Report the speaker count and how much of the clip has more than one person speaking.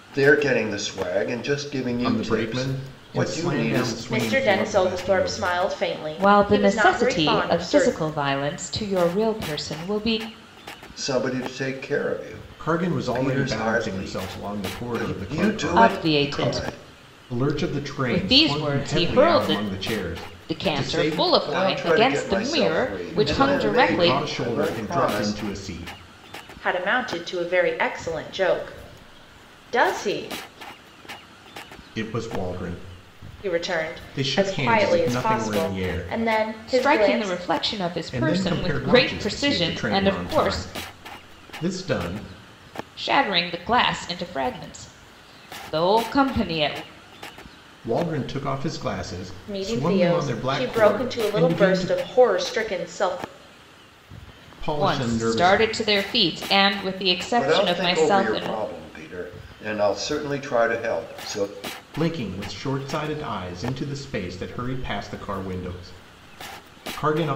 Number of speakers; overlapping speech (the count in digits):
4, about 41%